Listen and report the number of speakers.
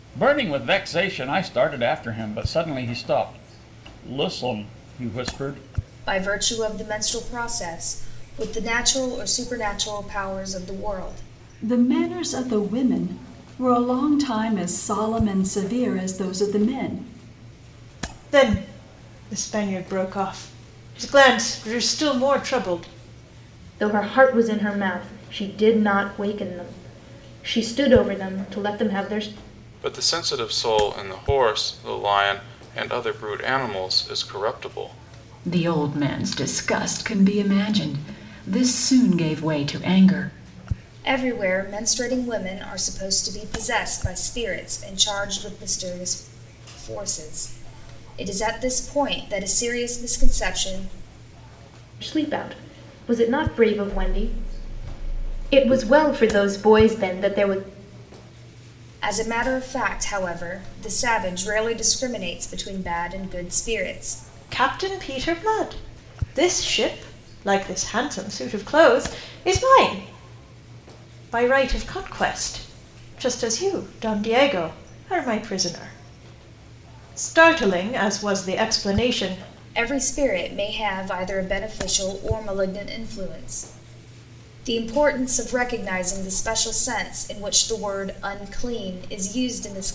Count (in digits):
7